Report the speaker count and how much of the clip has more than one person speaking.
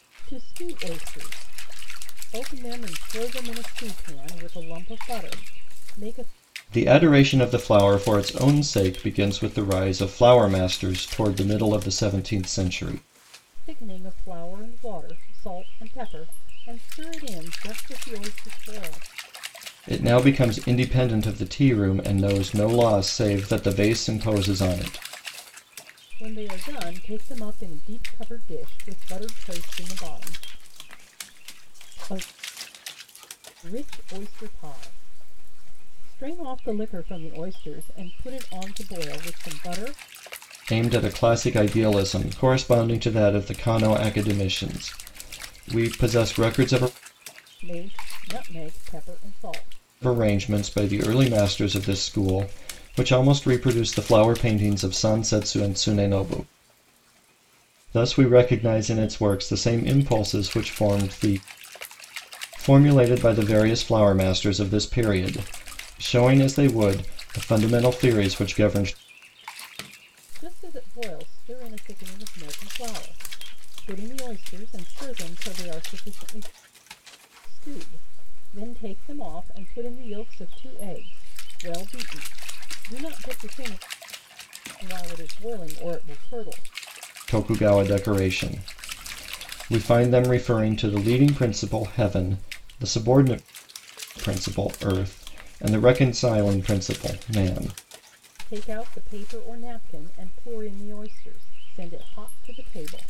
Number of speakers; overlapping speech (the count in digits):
2, no overlap